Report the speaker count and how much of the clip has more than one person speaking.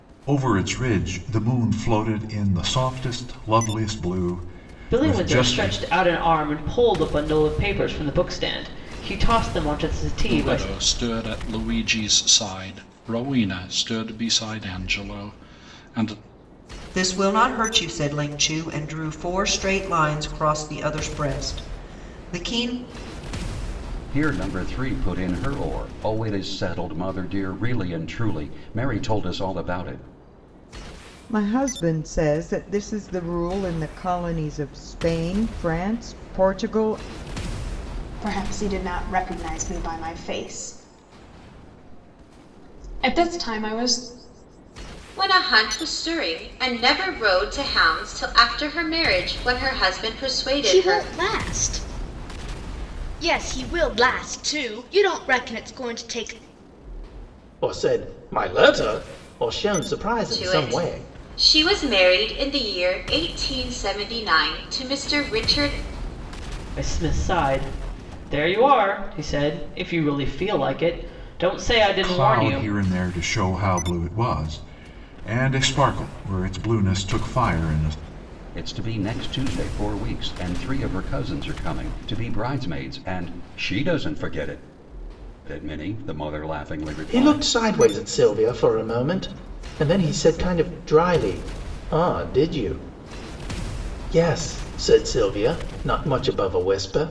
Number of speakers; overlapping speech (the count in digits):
10, about 4%